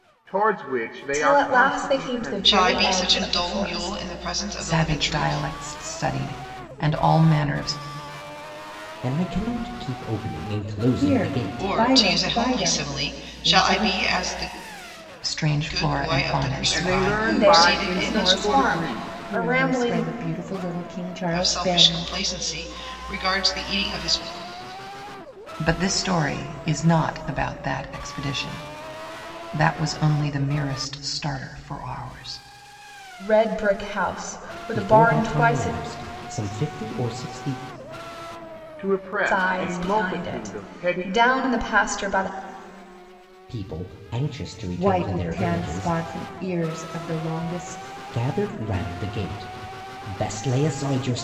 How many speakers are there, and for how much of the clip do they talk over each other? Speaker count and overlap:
six, about 32%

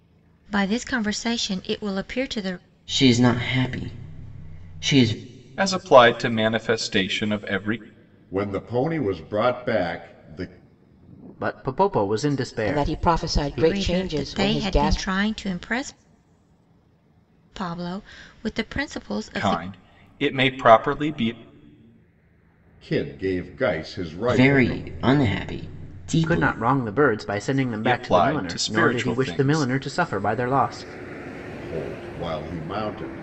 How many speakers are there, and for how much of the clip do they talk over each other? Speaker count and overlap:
six, about 17%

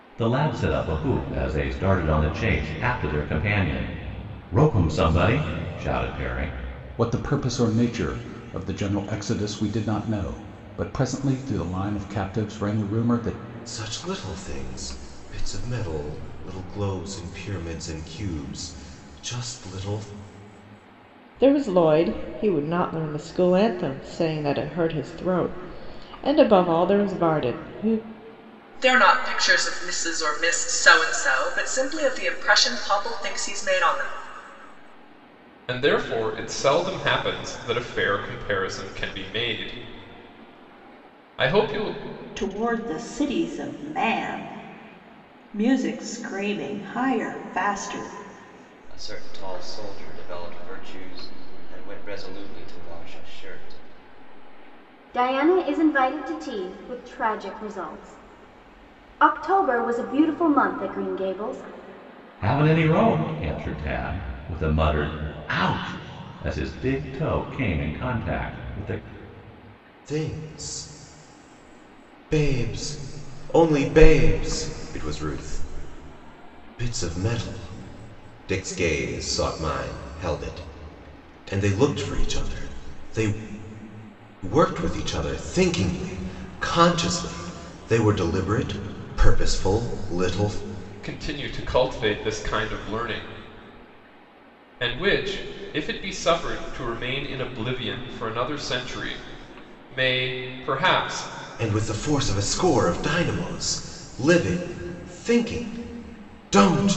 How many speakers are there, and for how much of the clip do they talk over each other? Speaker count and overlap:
nine, no overlap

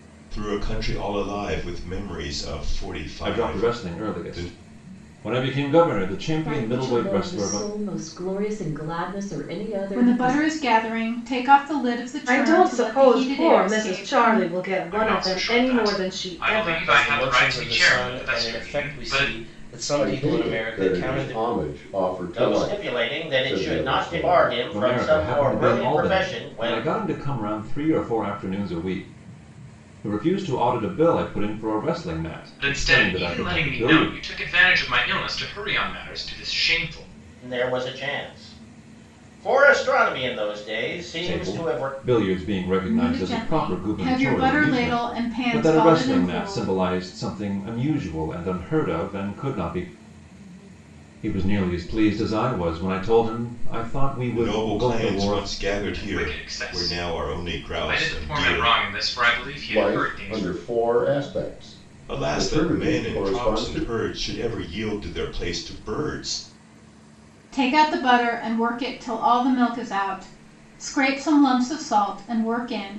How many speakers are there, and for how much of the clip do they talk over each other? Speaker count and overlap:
nine, about 38%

